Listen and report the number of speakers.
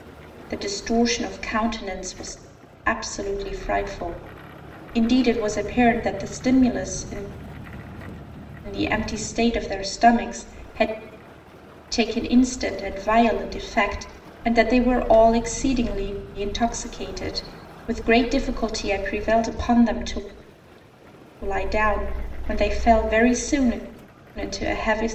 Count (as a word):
one